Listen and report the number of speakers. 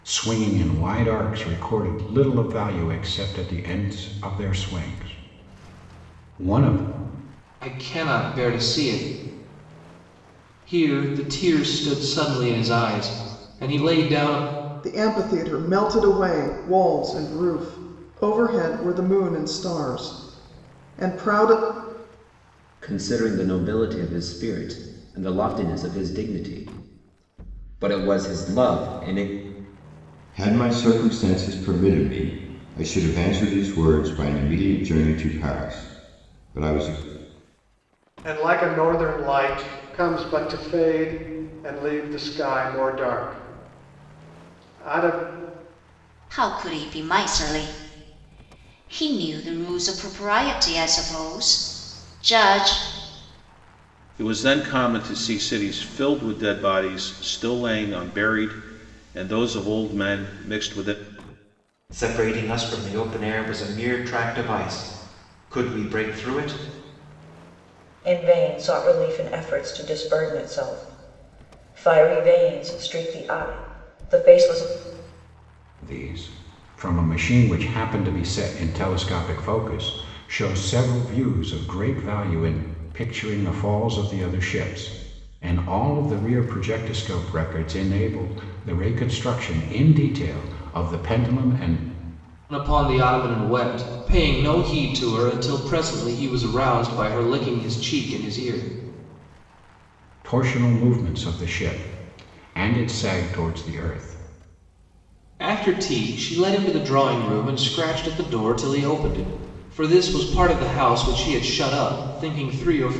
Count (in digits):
10